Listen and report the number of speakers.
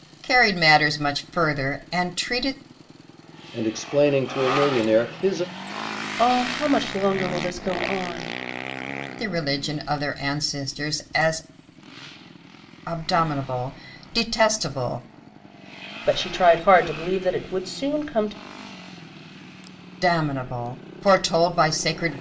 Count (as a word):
three